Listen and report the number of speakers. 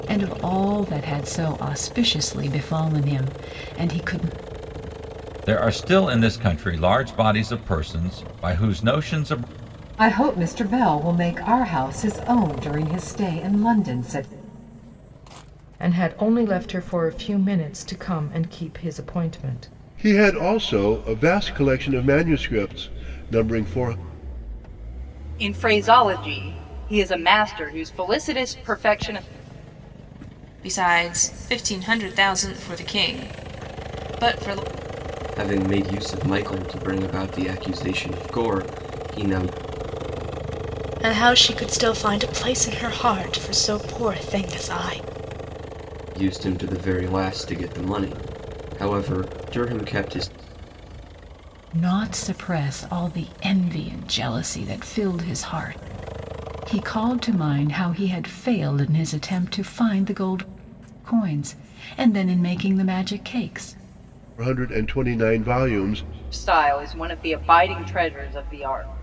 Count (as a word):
nine